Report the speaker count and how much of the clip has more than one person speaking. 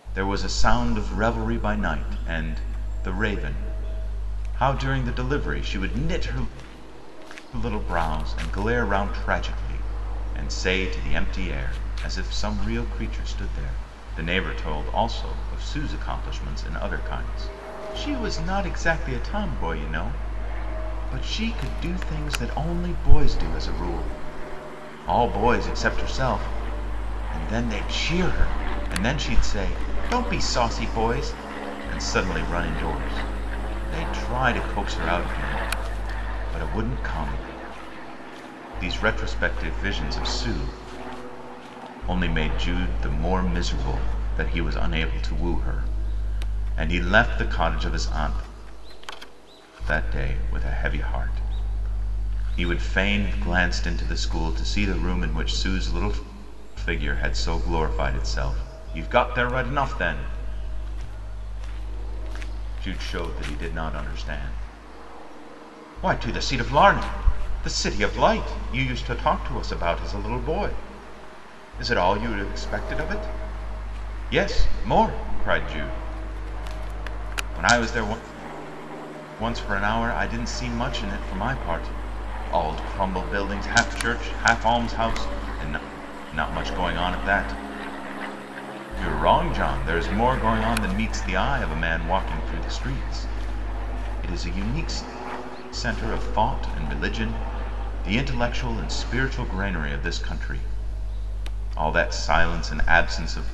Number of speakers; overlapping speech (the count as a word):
one, no overlap